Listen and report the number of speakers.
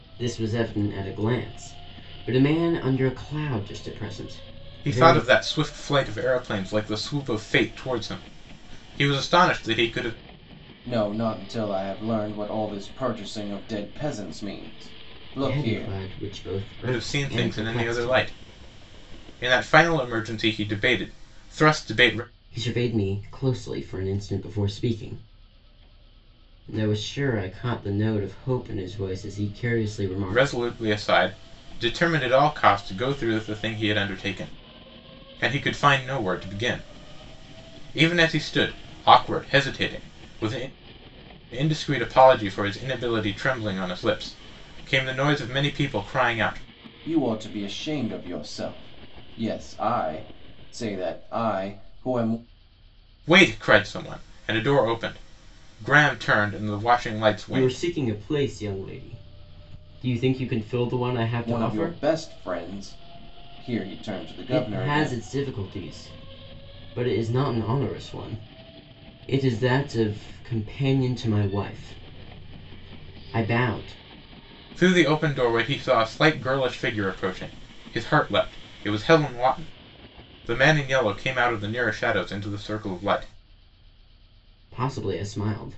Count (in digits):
3